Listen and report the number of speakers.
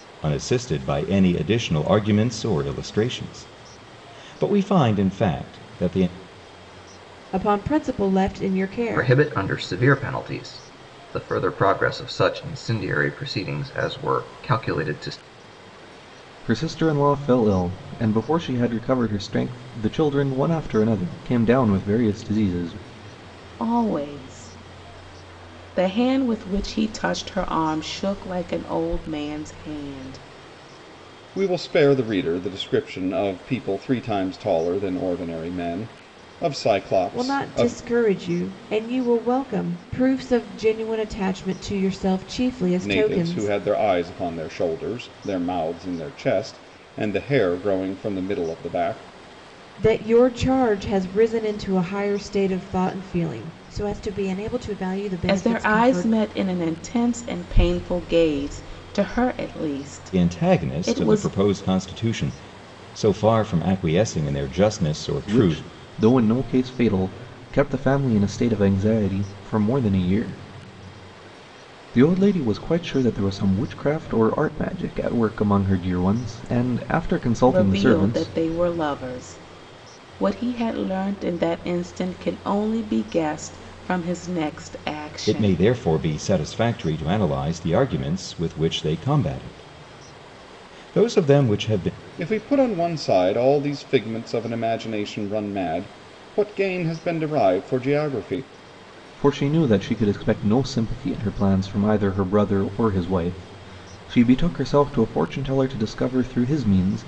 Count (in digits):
6